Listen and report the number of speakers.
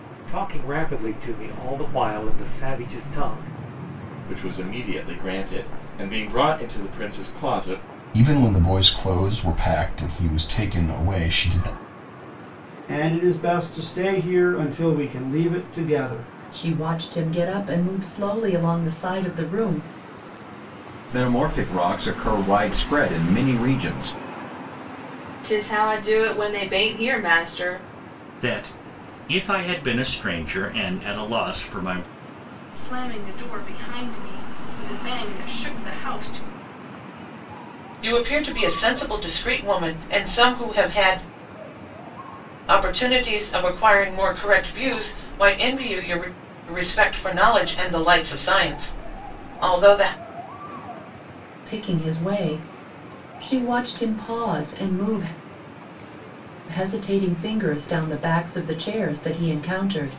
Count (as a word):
ten